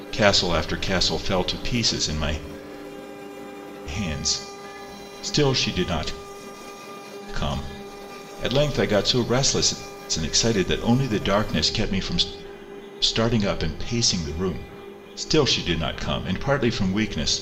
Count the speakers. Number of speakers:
1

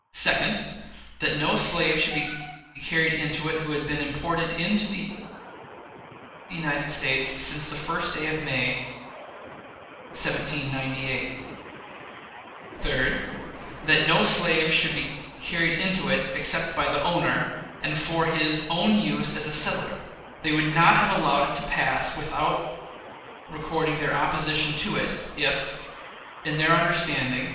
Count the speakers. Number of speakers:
1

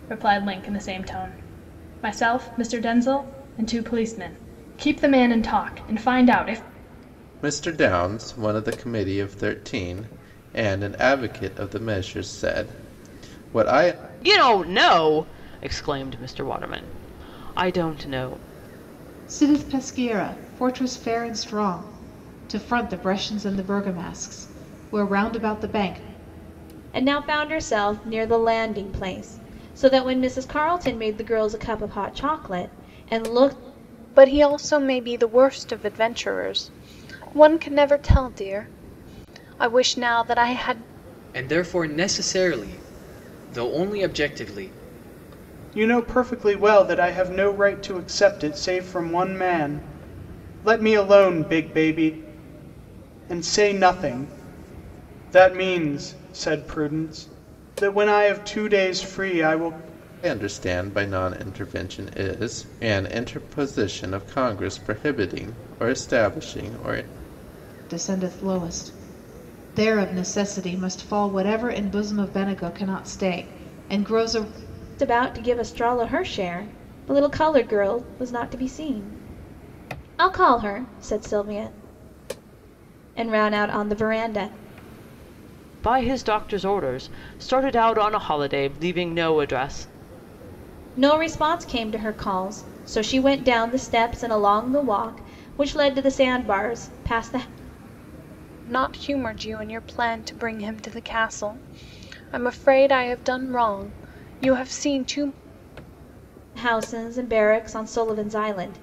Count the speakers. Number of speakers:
8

